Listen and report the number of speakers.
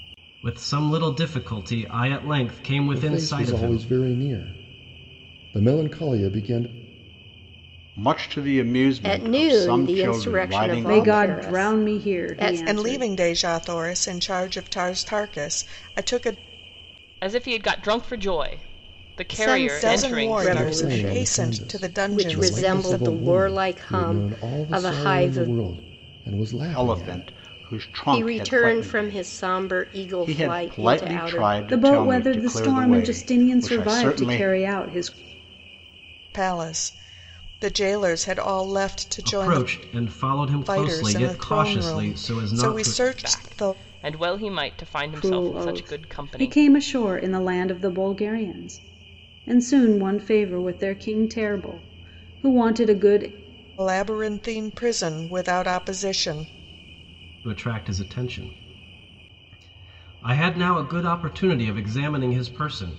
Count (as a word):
seven